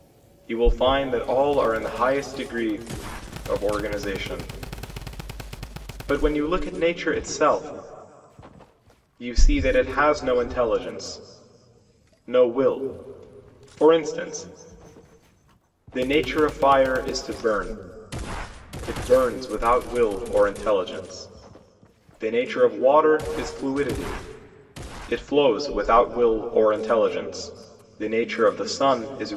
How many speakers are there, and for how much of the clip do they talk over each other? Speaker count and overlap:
1, no overlap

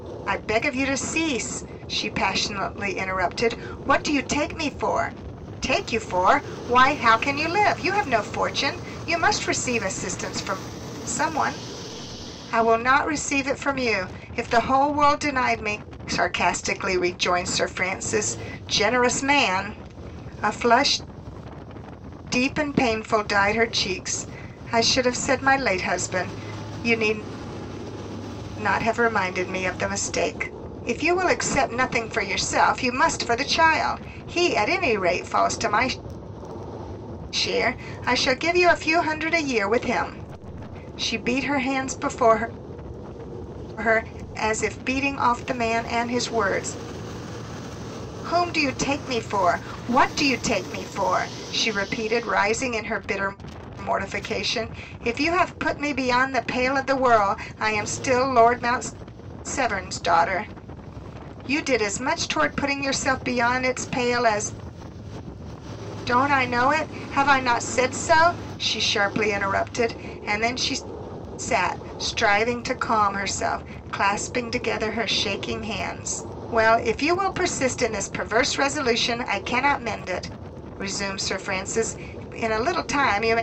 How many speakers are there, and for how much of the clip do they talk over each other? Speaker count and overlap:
1, no overlap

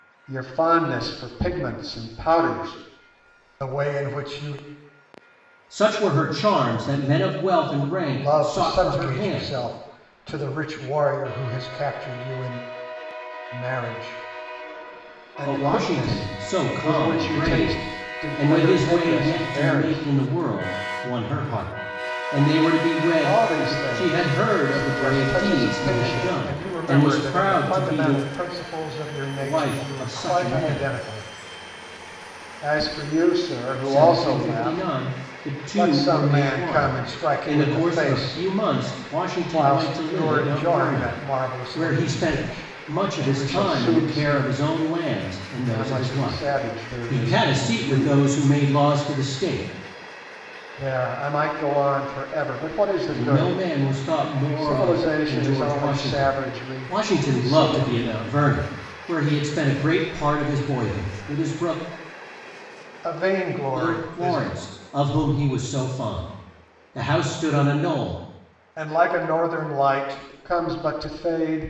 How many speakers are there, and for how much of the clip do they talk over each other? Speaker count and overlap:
2, about 41%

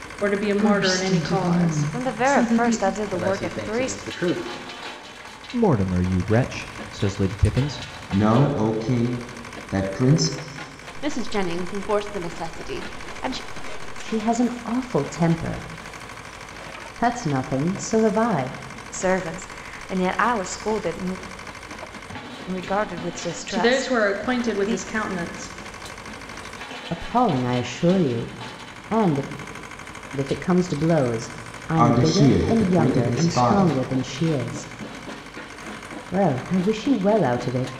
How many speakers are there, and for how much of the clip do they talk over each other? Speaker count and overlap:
8, about 17%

